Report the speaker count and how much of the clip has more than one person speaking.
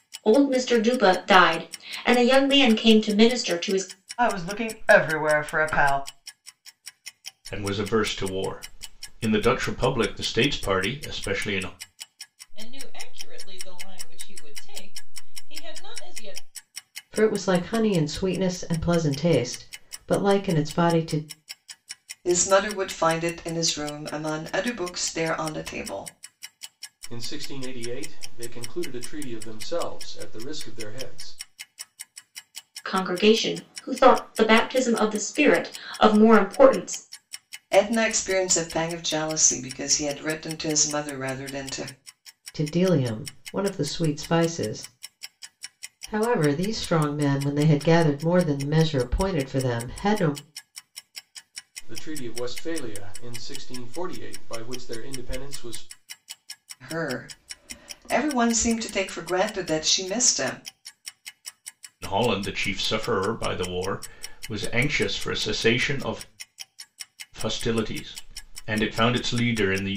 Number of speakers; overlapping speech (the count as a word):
seven, no overlap